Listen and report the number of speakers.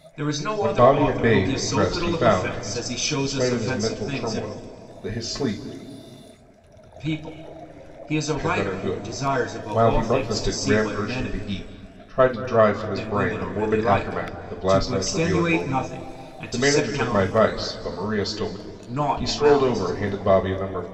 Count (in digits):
2